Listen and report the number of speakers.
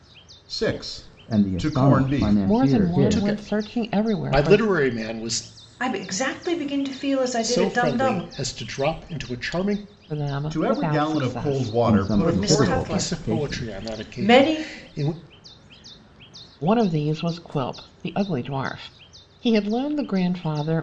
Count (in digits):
5